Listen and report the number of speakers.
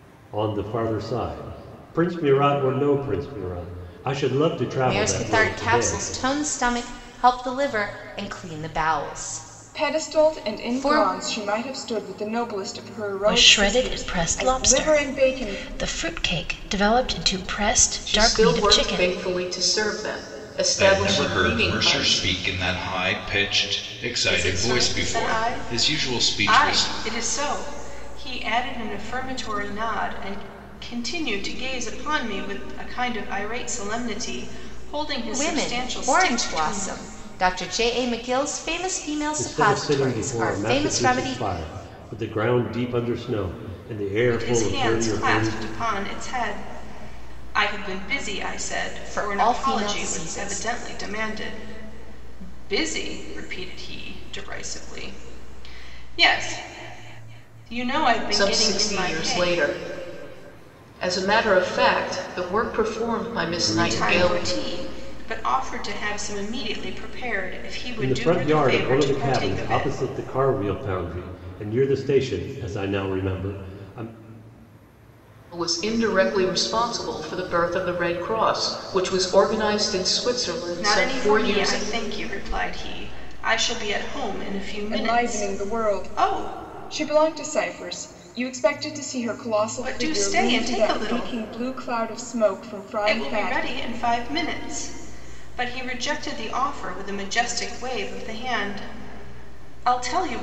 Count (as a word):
seven